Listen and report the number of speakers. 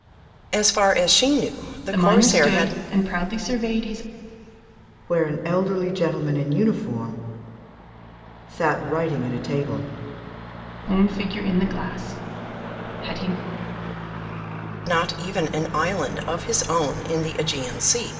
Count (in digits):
3